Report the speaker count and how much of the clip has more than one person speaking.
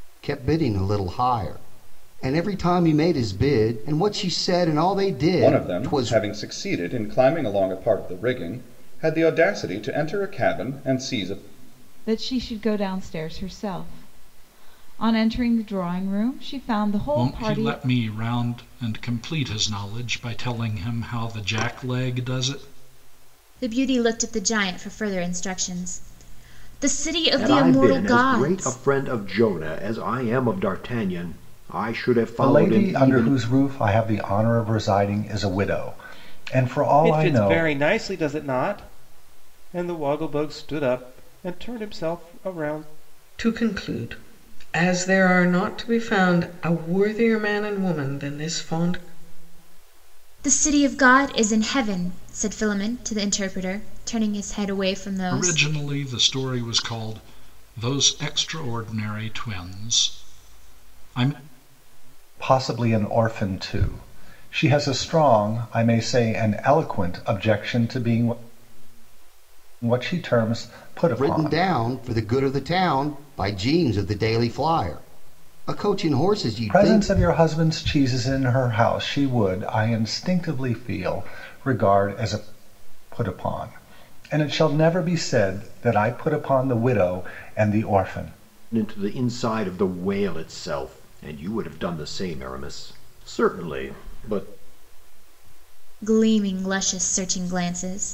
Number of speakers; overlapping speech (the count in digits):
9, about 6%